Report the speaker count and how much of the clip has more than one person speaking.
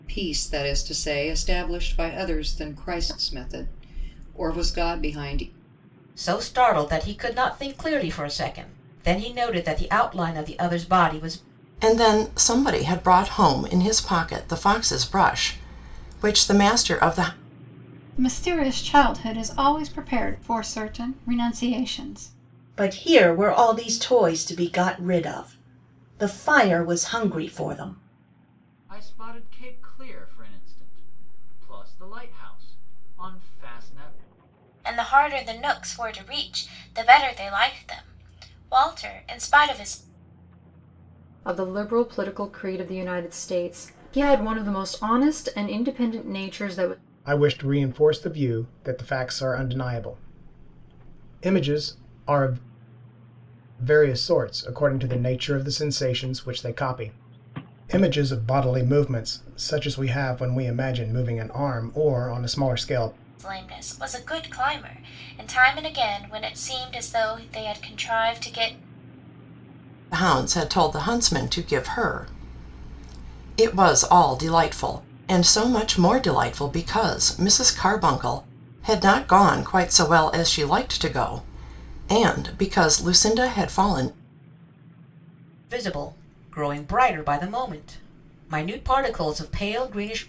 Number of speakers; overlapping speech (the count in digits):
9, no overlap